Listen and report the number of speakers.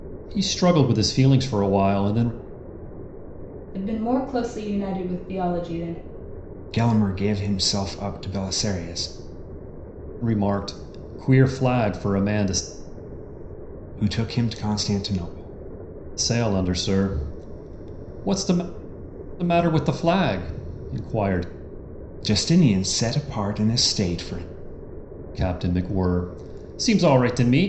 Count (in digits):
3